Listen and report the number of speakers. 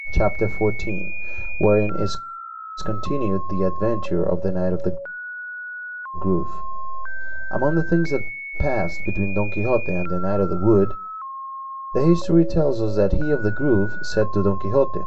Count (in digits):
1